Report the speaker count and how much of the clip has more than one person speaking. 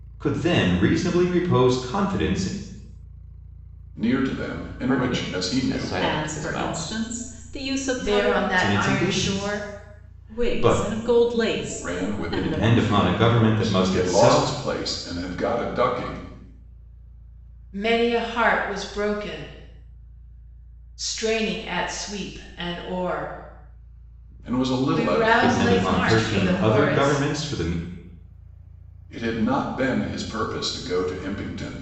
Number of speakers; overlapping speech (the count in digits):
5, about 30%